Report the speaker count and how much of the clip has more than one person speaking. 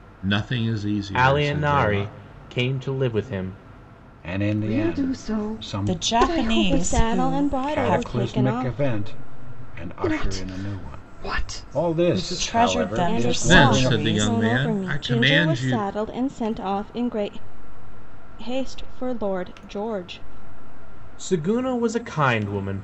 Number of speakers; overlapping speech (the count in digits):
6, about 47%